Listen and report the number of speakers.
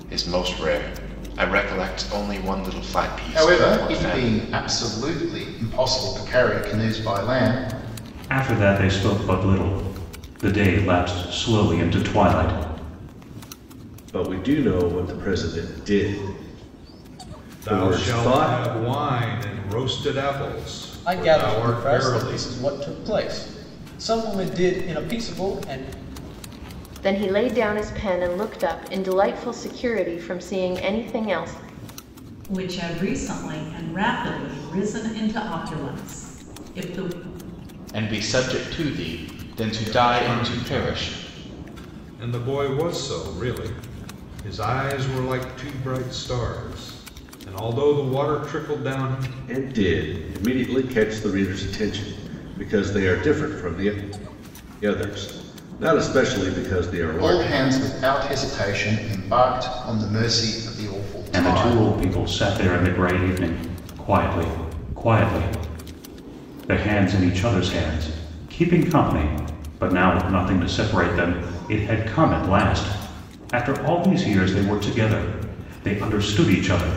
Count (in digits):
9